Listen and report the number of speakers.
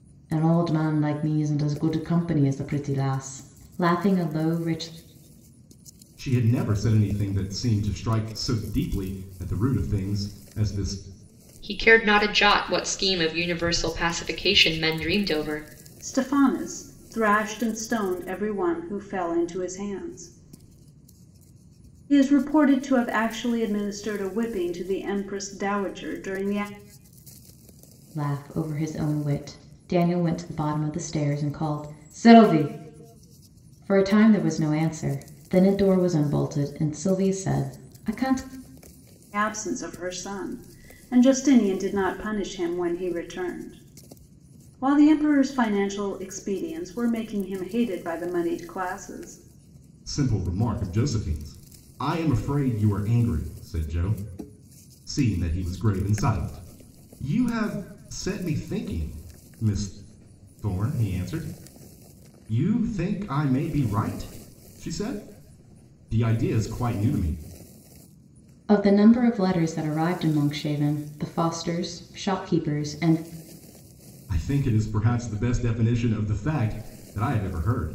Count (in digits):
4